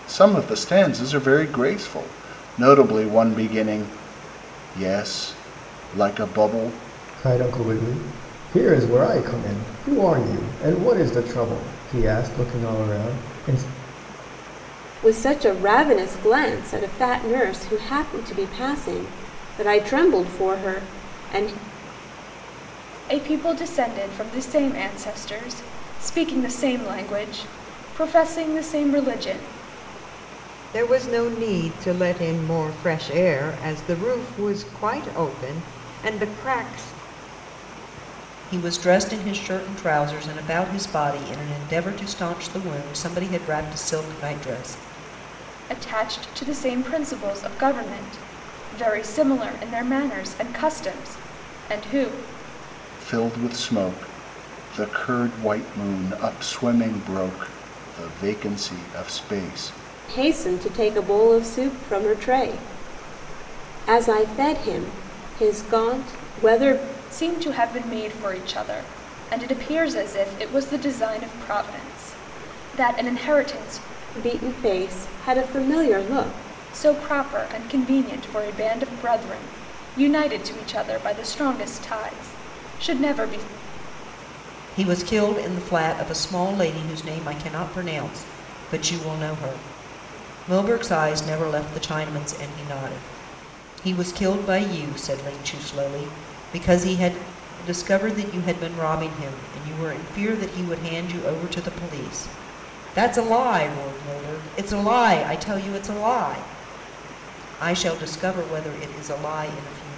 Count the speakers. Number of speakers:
six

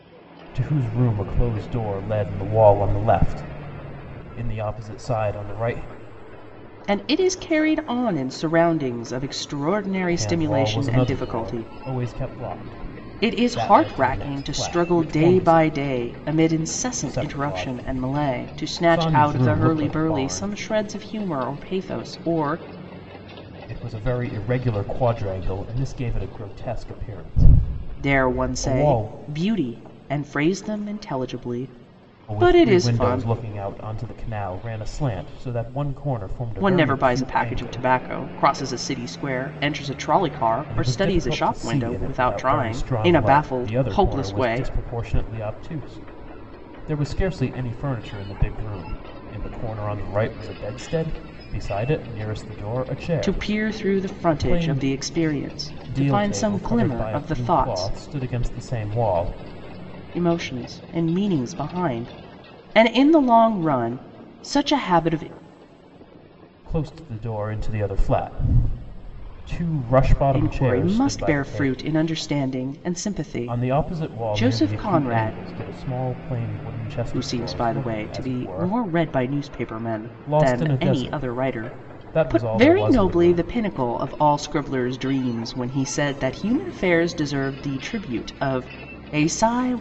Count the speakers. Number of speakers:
two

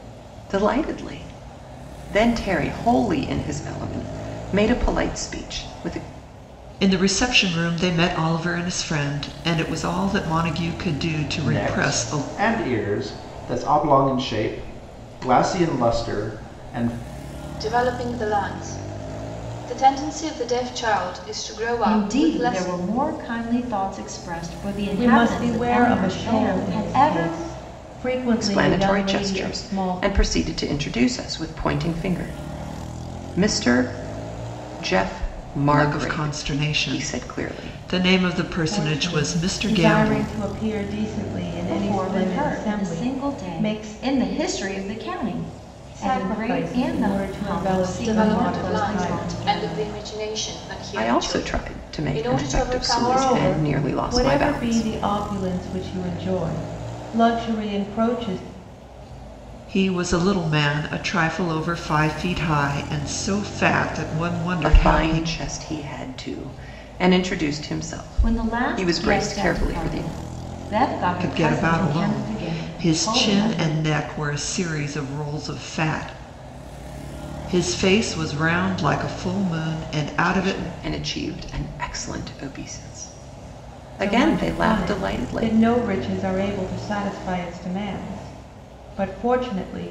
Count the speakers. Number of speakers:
six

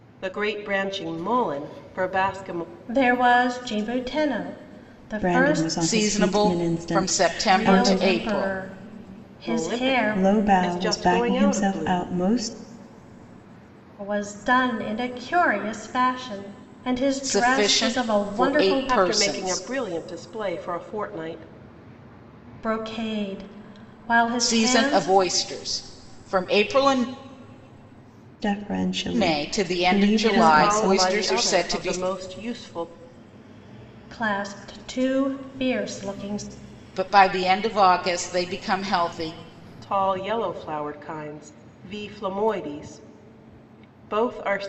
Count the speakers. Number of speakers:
four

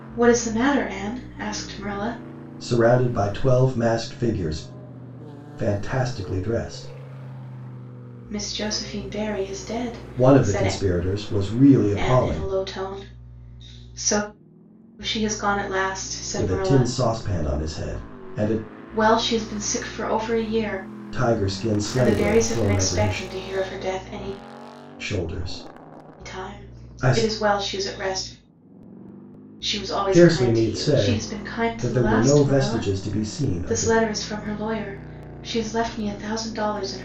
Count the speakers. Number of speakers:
two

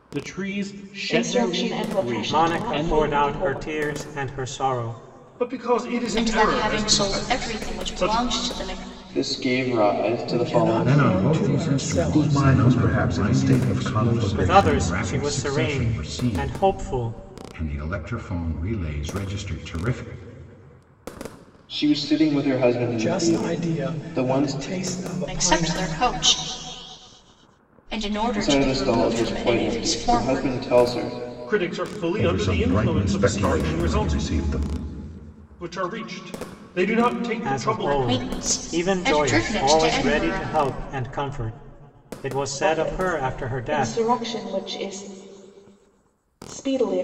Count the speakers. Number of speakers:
nine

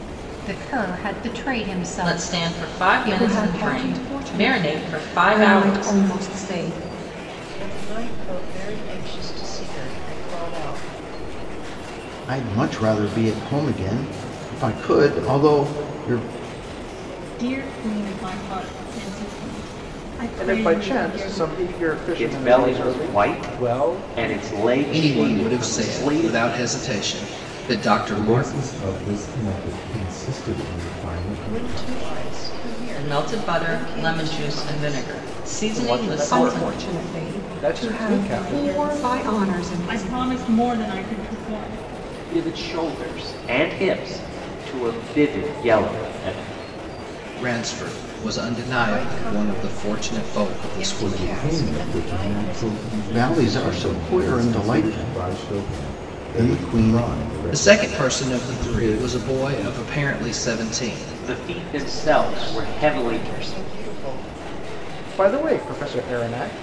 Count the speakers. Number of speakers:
ten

